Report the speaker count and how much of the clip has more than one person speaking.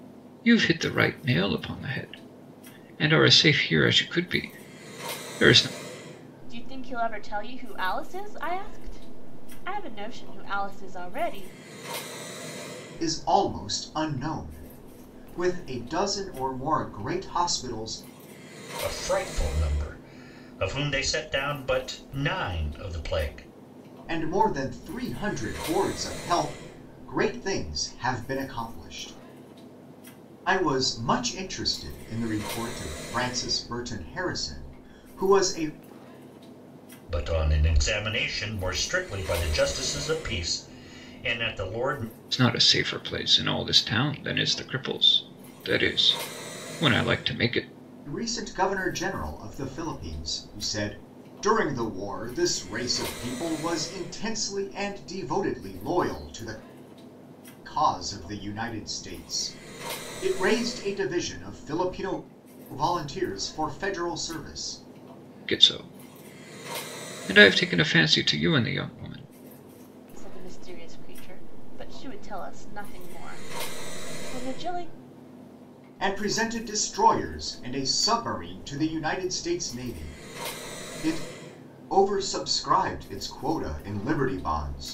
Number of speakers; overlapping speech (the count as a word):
four, no overlap